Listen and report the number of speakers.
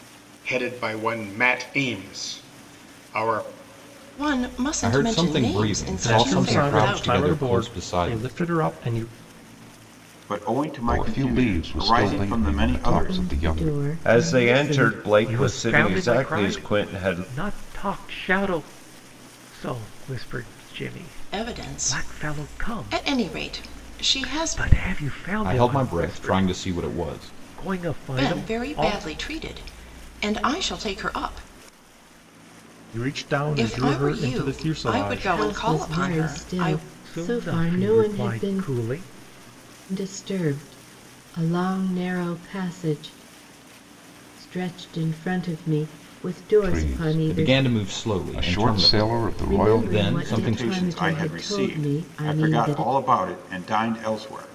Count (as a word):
nine